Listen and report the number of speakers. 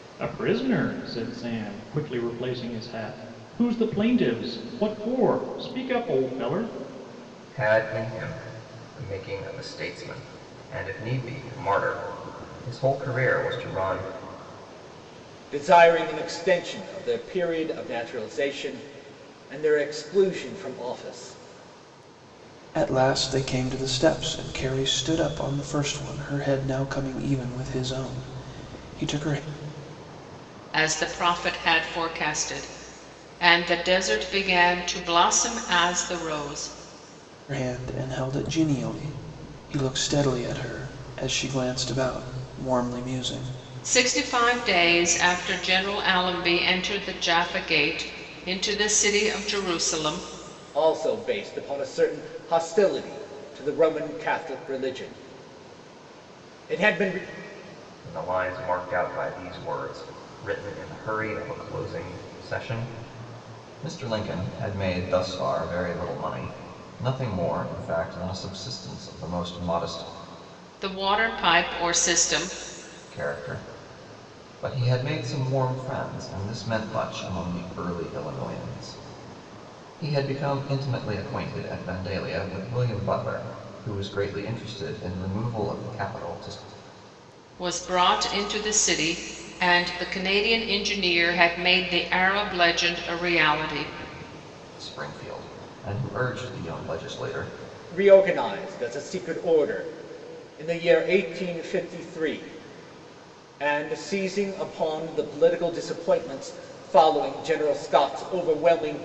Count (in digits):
5